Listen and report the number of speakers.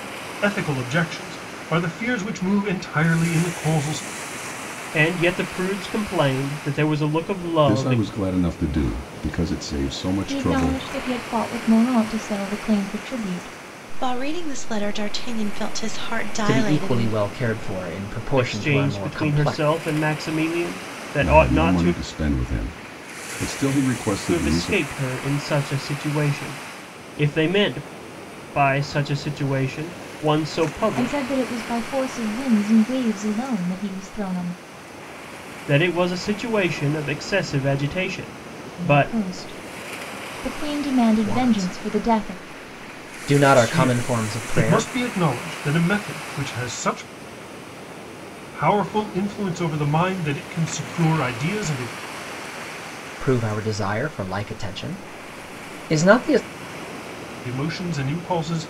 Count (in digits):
6